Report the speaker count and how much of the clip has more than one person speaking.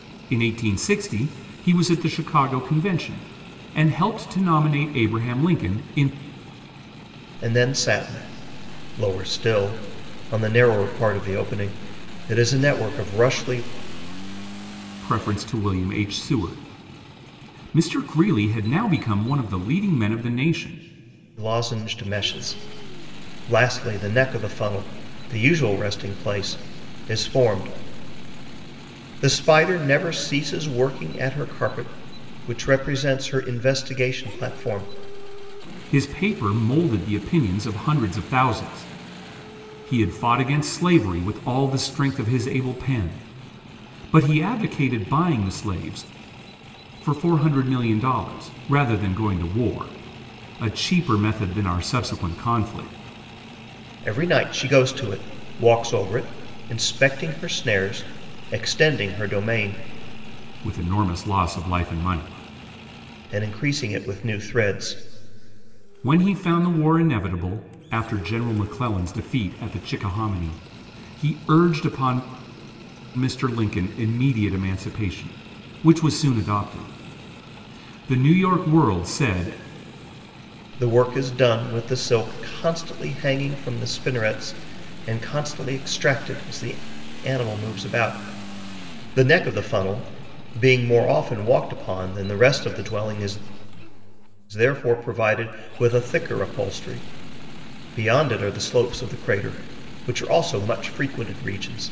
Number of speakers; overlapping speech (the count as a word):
two, no overlap